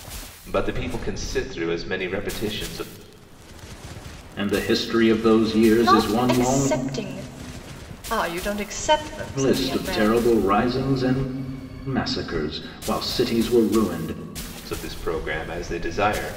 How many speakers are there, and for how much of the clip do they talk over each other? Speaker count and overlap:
3, about 11%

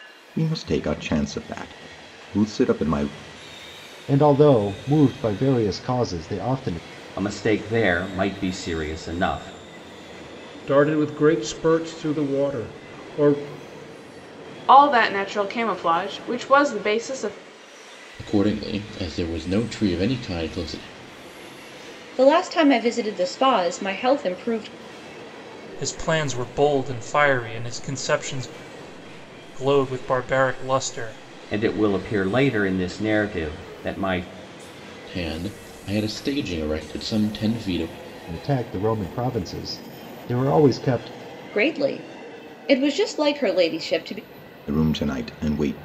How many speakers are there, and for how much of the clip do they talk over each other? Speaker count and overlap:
8, no overlap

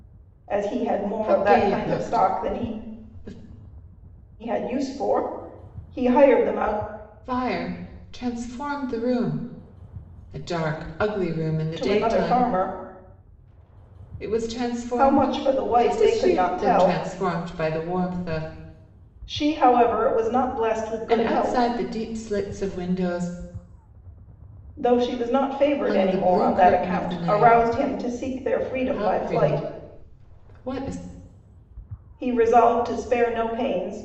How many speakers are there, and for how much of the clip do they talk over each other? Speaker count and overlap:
2, about 23%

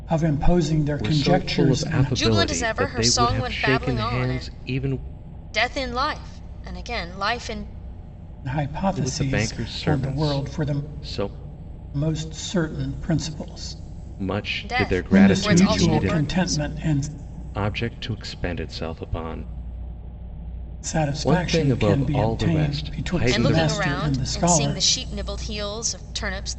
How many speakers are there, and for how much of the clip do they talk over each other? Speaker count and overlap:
3, about 42%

